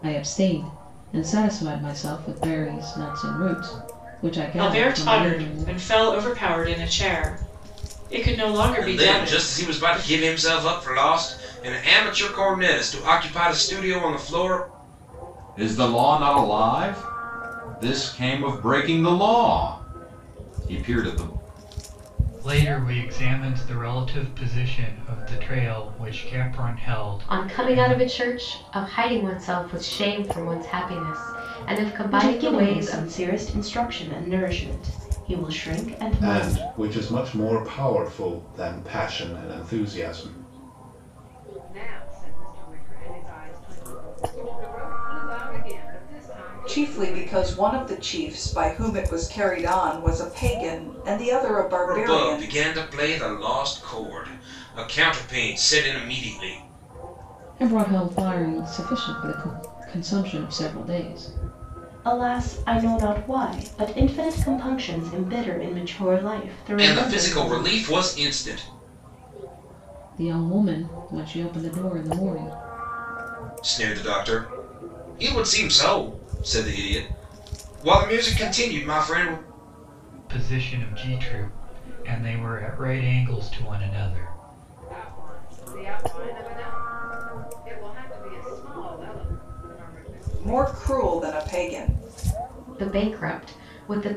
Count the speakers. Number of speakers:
10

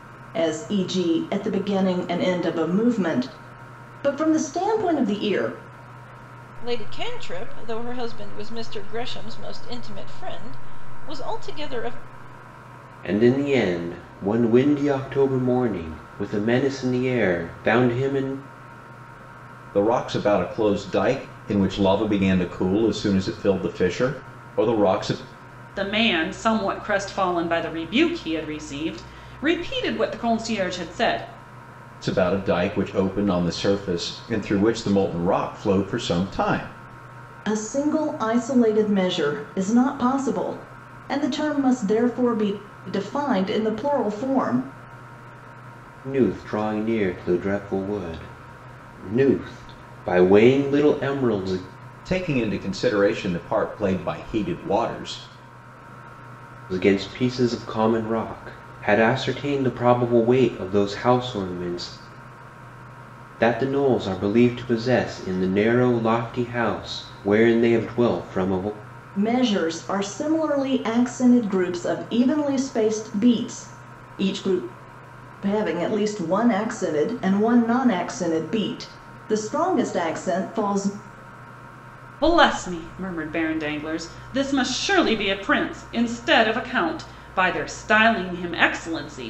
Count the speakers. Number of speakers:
5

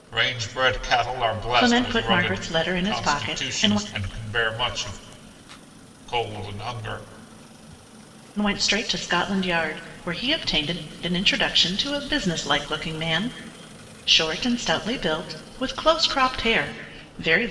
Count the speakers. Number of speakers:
2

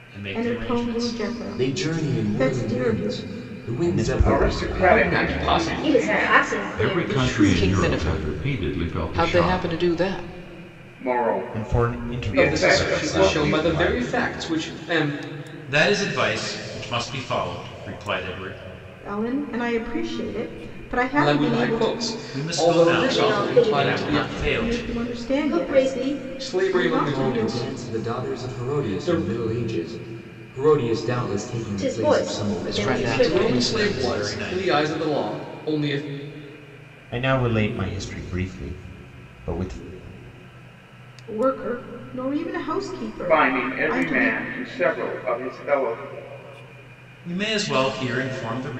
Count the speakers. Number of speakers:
9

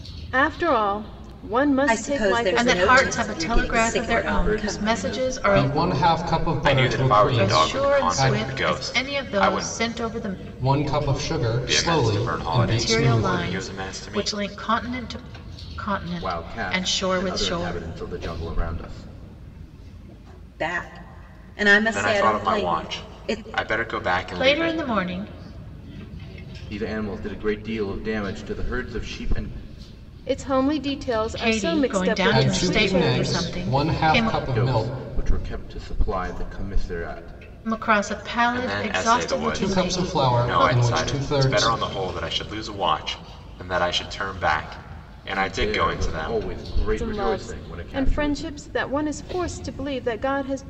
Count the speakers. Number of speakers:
6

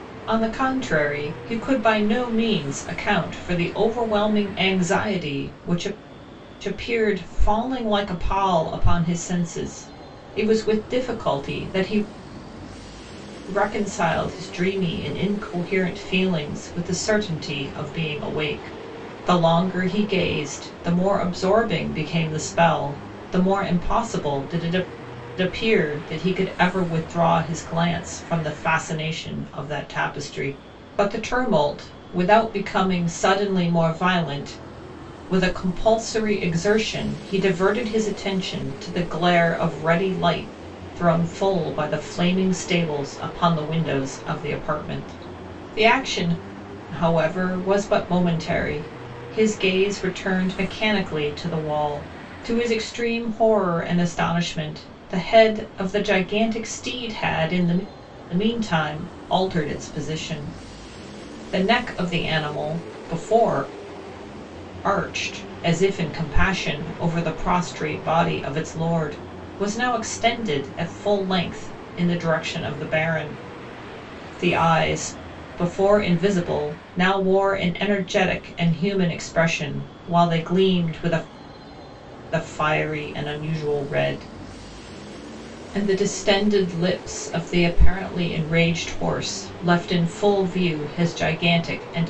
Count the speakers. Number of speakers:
1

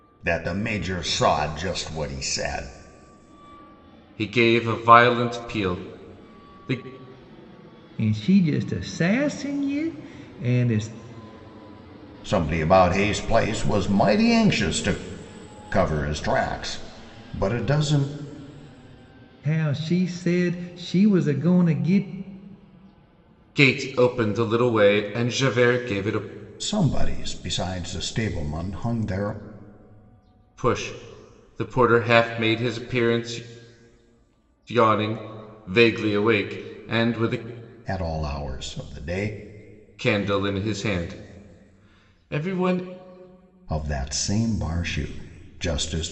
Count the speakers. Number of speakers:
3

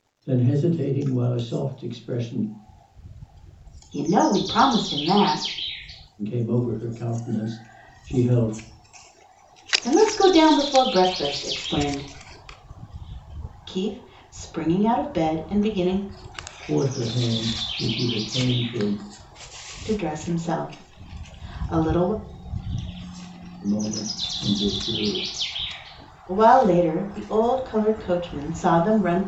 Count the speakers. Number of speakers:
2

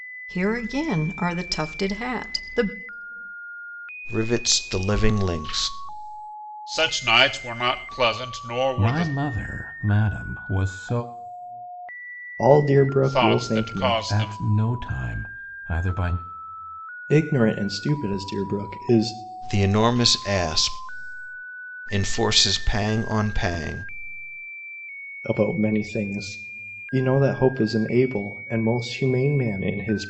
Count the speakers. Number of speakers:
5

